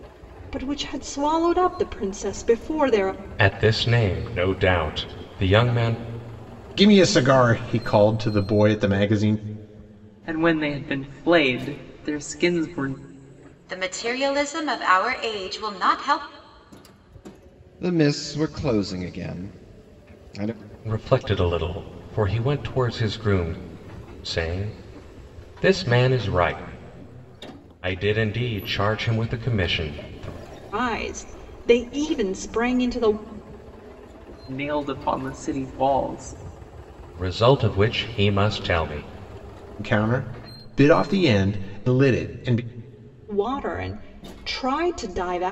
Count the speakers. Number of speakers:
6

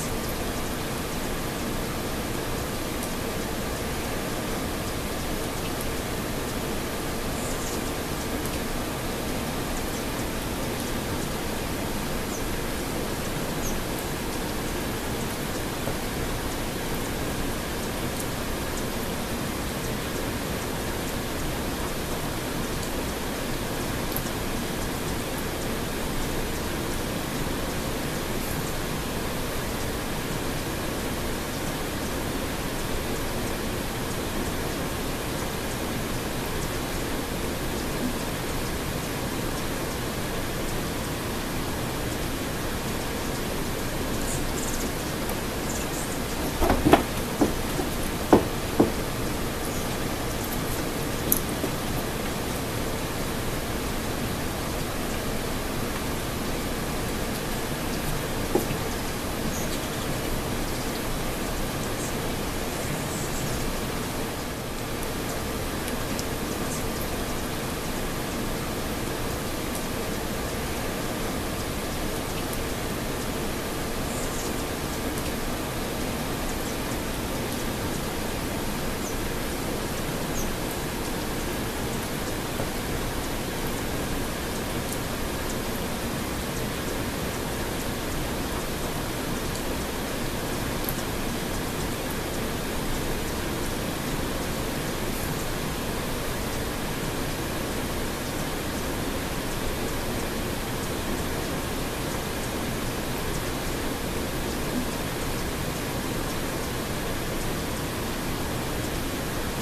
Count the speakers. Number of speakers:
0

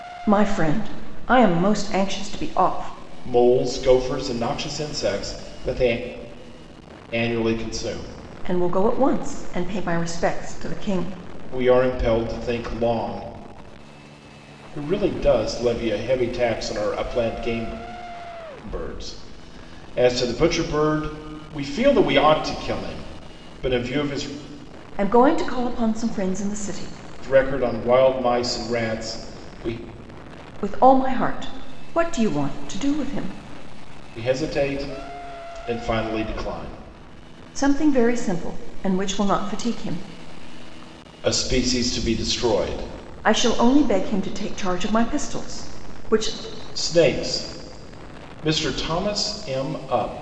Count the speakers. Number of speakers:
2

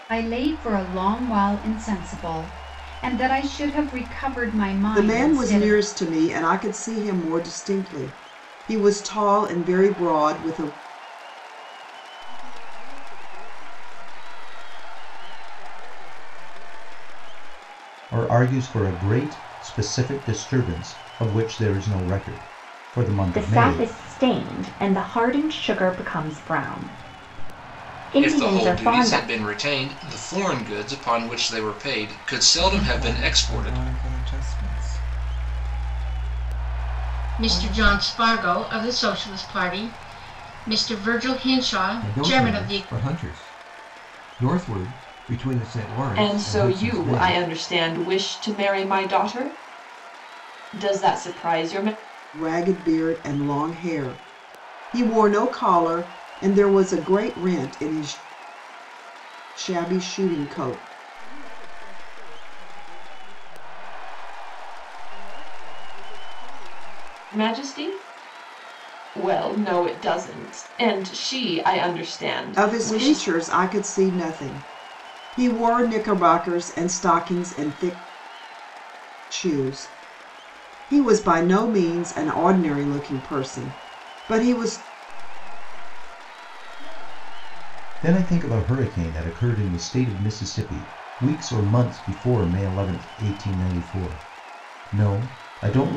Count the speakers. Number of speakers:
10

